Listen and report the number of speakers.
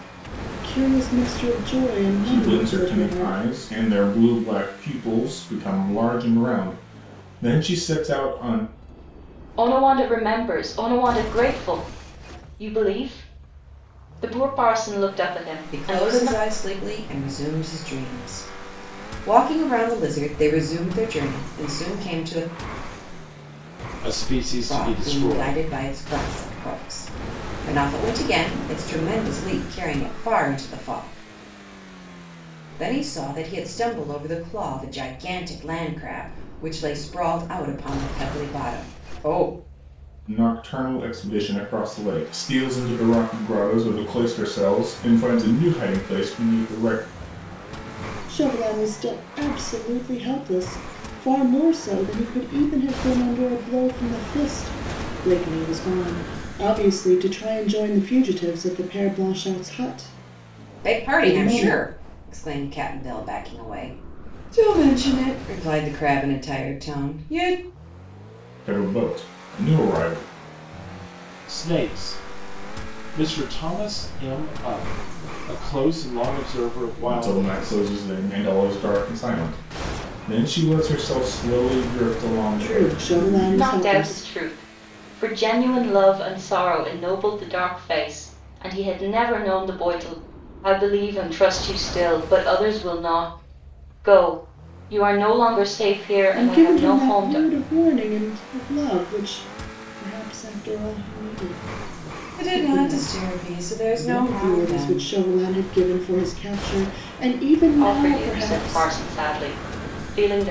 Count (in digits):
5